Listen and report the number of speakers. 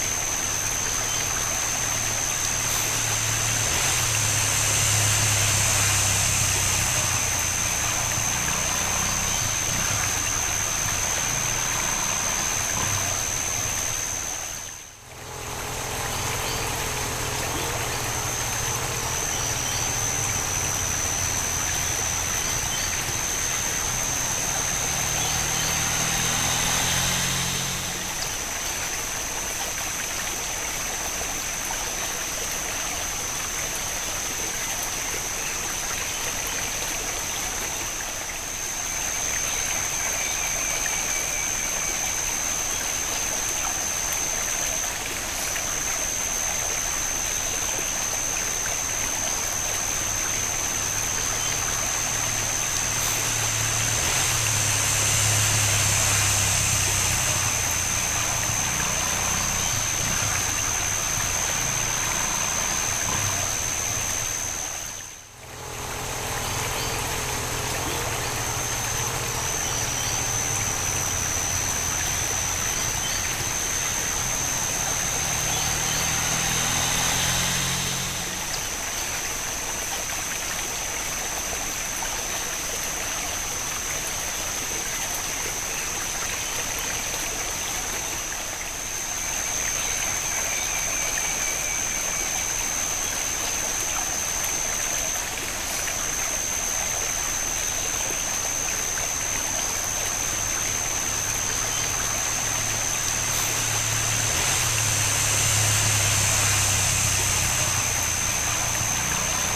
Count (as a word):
zero